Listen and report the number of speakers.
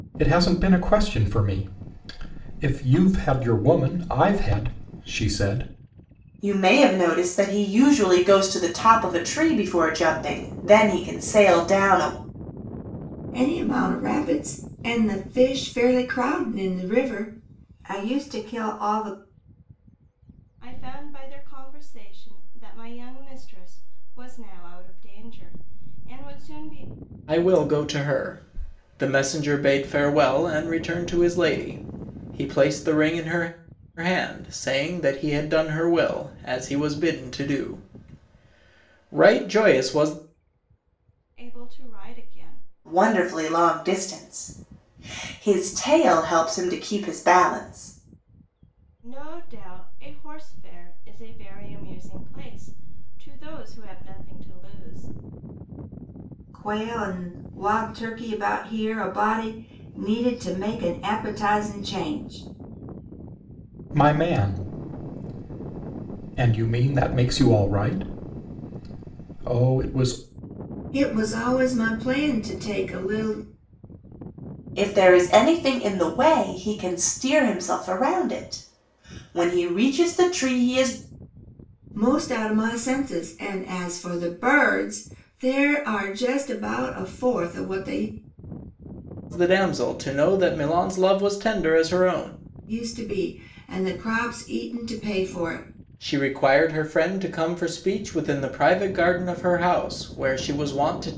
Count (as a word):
five